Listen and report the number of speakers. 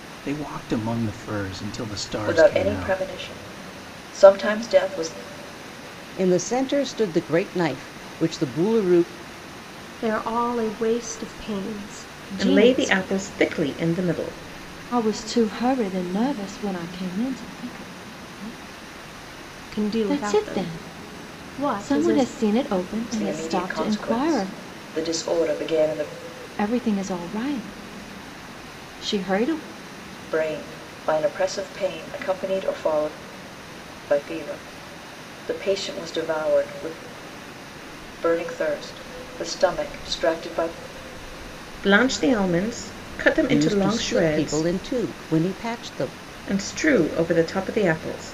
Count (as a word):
six